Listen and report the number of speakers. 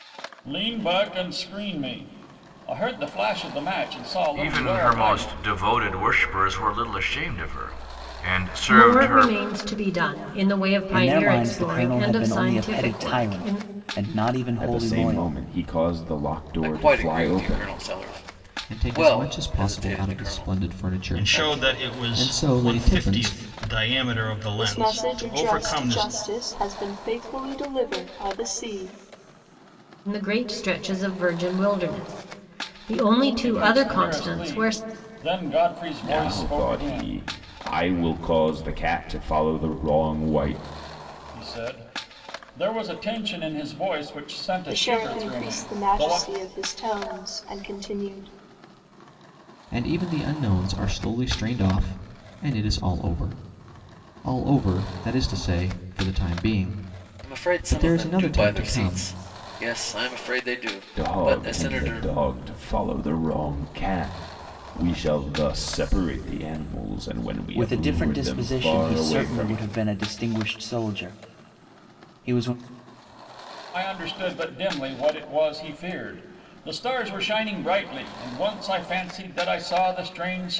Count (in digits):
9